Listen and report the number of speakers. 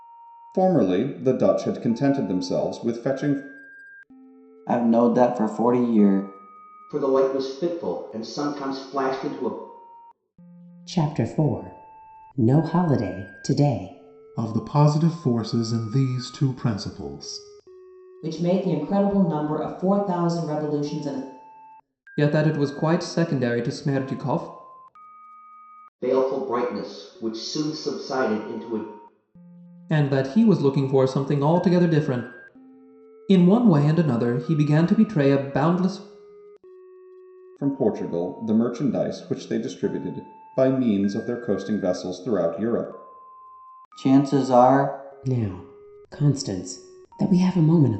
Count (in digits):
7